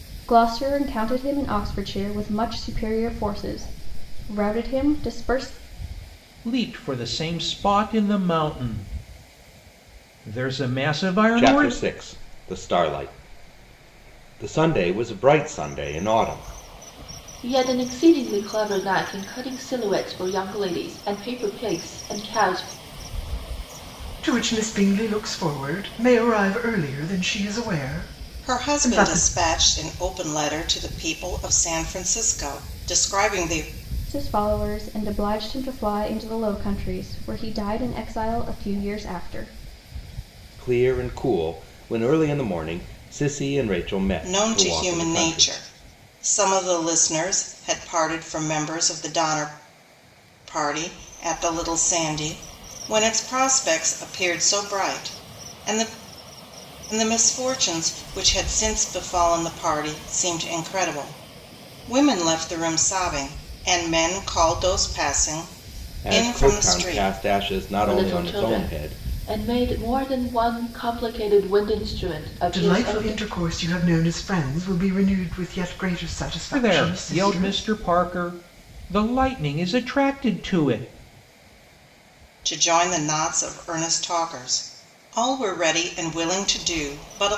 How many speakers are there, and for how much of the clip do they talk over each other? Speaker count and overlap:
6, about 8%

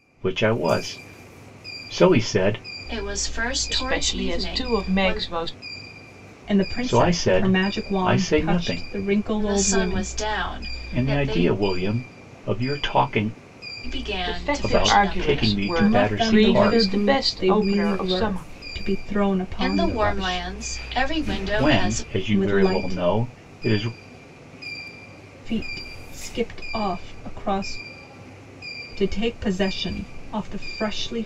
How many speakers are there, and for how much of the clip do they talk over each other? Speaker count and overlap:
4, about 38%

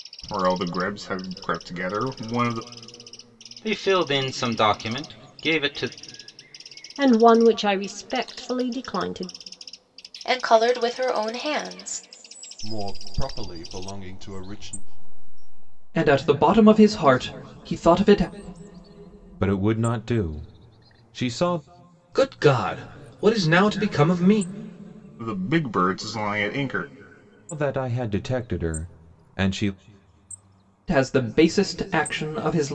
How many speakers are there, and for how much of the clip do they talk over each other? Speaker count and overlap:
8, no overlap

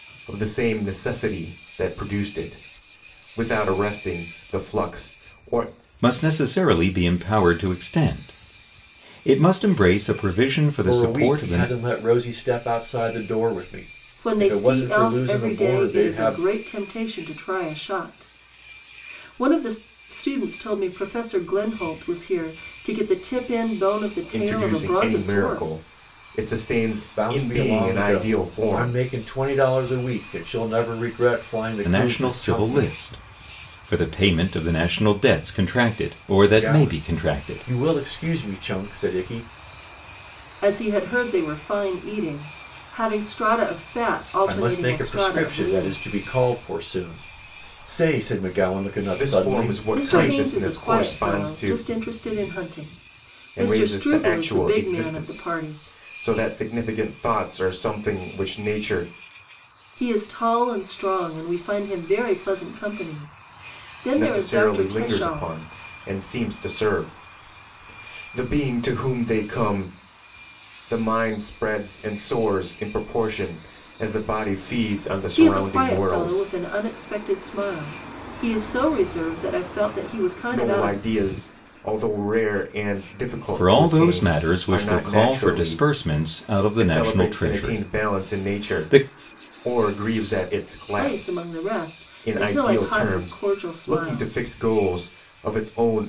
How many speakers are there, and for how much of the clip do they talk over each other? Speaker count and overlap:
4, about 27%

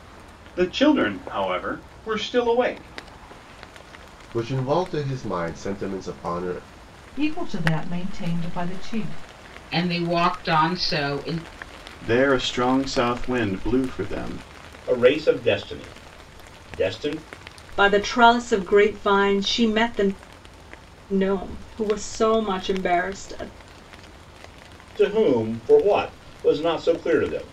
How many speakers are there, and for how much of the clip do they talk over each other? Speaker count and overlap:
7, no overlap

